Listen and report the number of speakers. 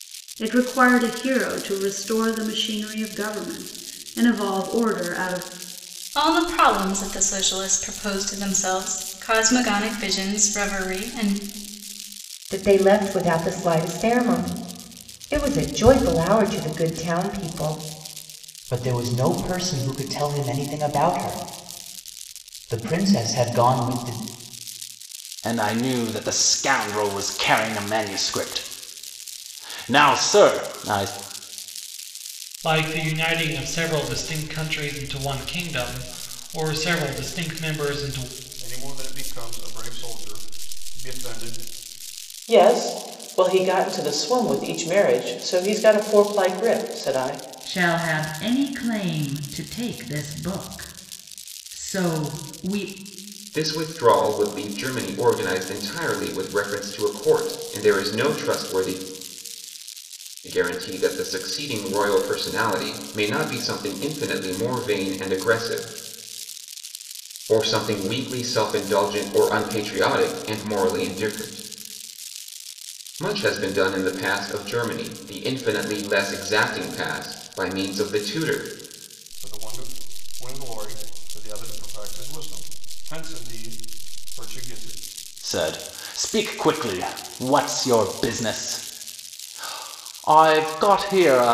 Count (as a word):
ten